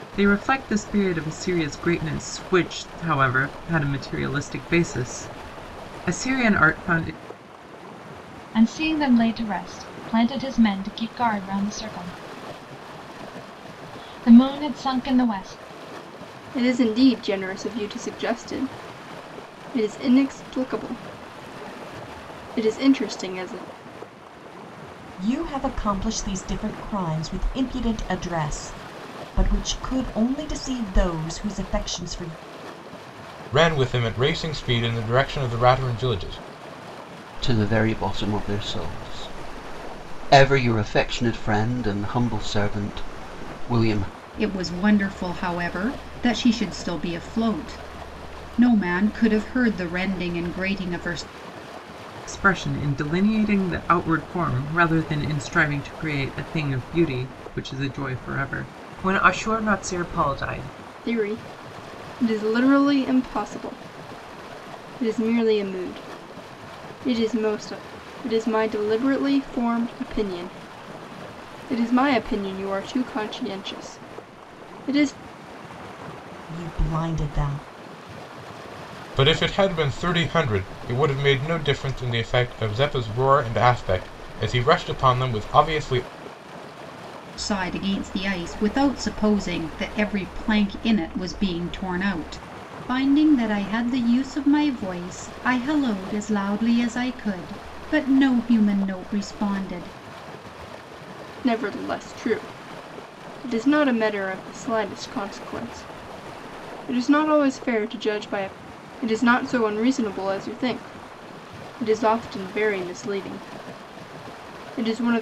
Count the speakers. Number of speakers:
seven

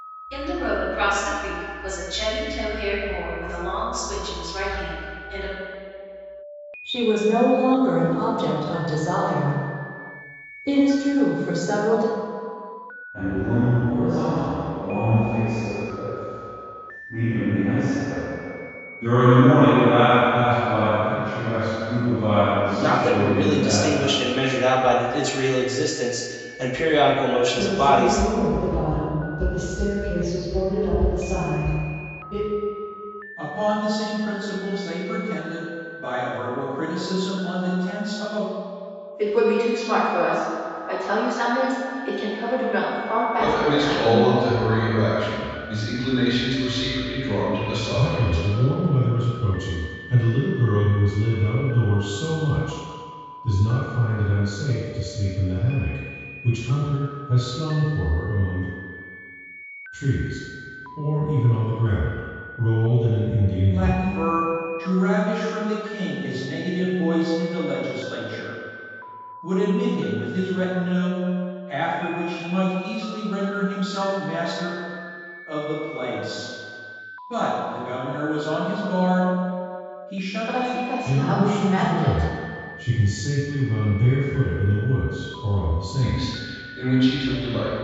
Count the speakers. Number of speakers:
ten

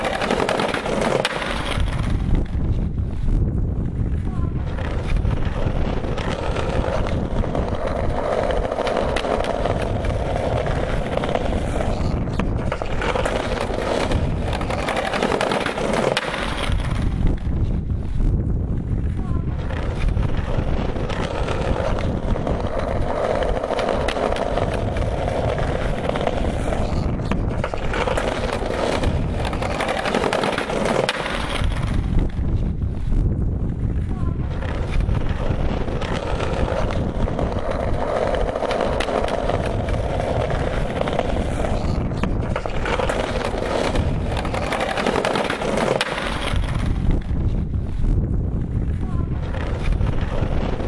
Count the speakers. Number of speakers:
zero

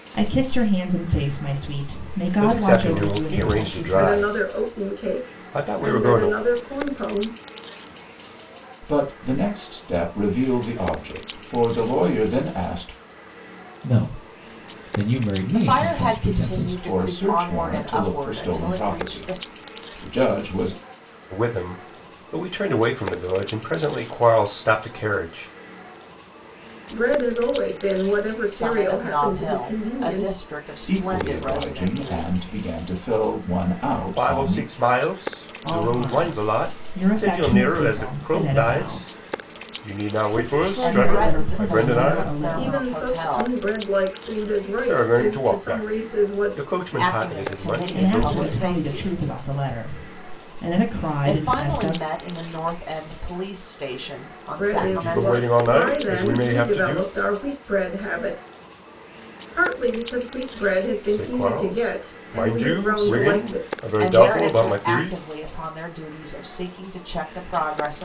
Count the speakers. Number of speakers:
six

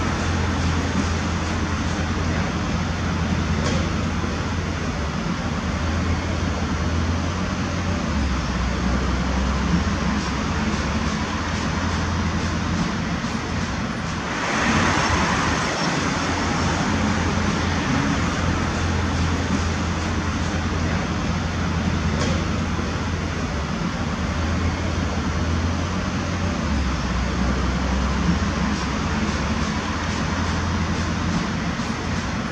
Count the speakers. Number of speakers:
zero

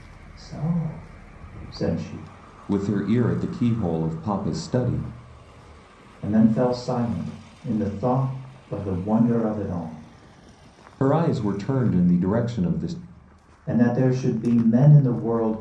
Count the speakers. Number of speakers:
two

